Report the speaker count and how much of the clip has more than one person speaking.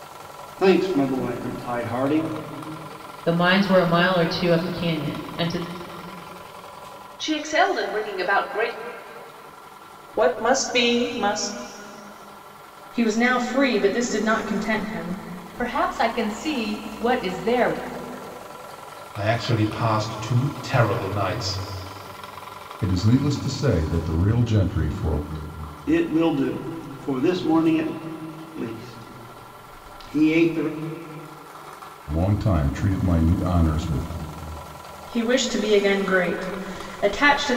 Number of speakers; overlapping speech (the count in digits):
8, no overlap